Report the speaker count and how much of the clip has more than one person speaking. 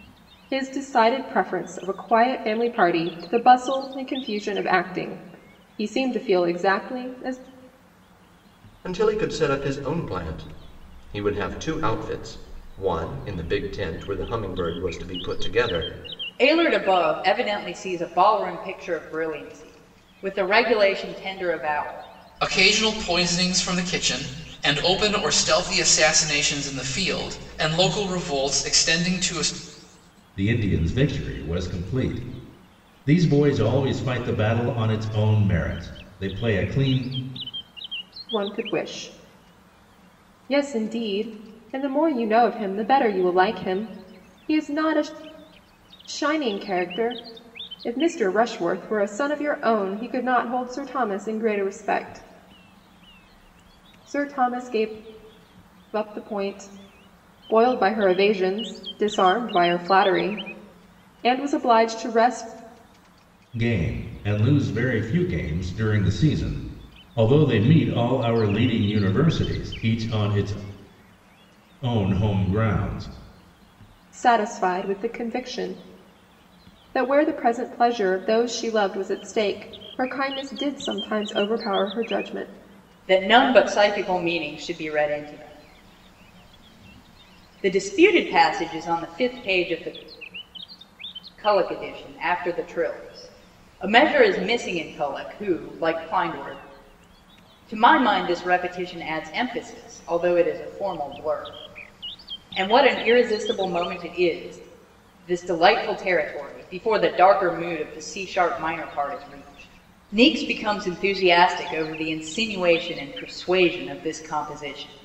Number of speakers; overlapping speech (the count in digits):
5, no overlap